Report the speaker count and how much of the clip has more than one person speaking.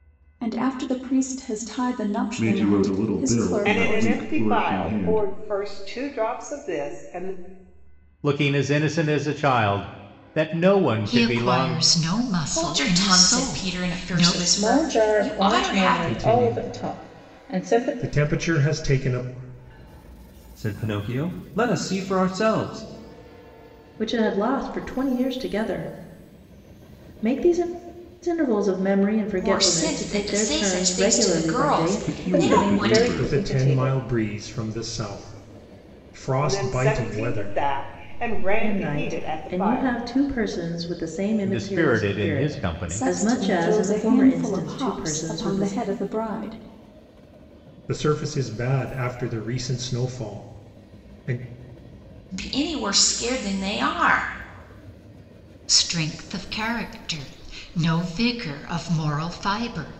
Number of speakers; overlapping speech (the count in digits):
10, about 35%